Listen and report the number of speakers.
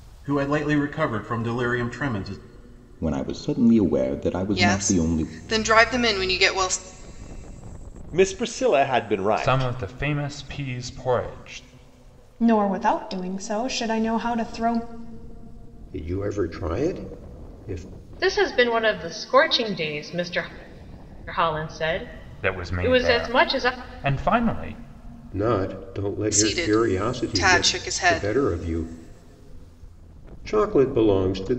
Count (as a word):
eight